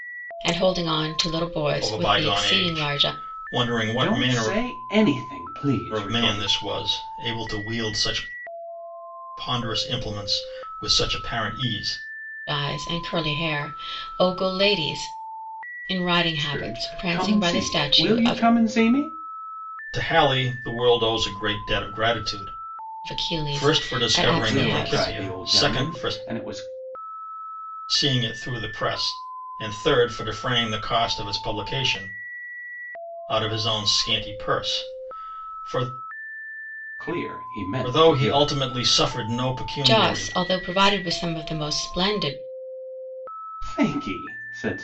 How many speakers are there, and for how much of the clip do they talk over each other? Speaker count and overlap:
three, about 19%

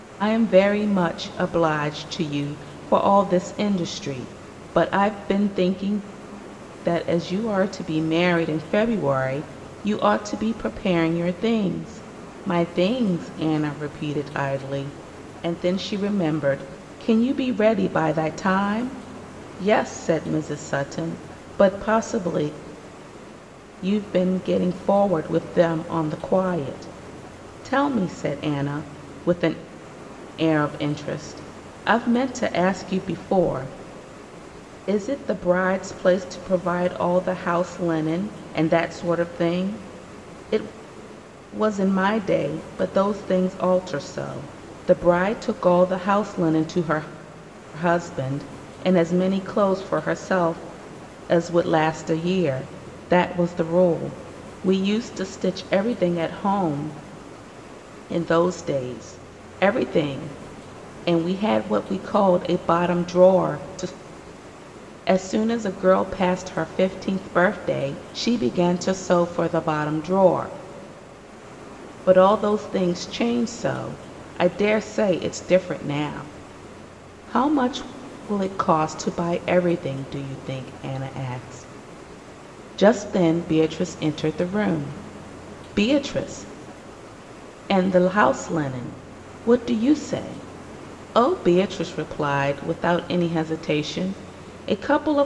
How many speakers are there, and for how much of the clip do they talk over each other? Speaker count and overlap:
one, no overlap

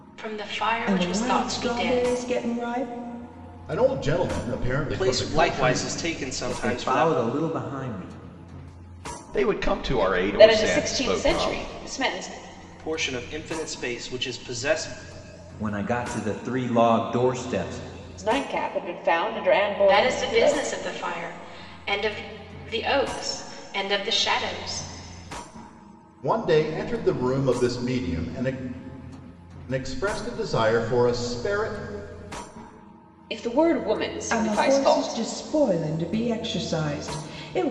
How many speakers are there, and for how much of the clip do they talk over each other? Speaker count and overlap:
seven, about 16%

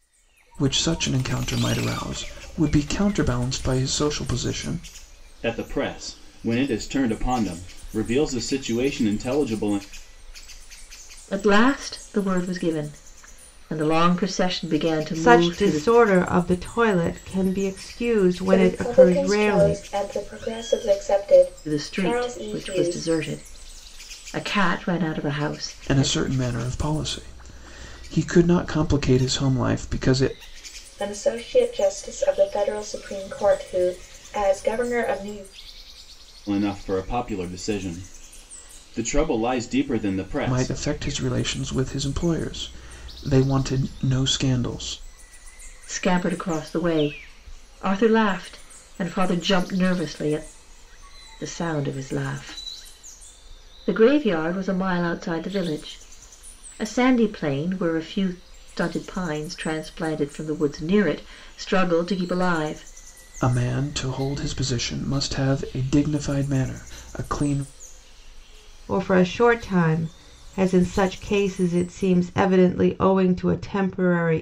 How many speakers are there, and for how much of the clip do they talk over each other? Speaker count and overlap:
five, about 6%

